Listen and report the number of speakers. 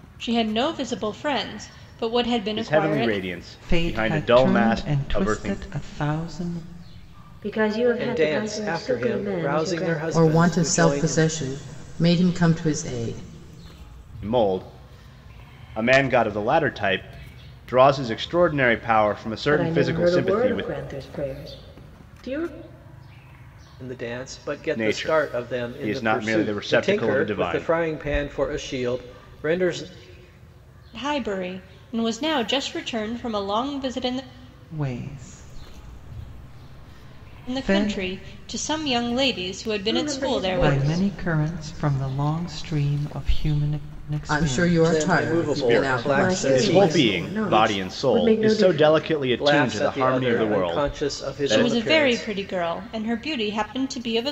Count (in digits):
6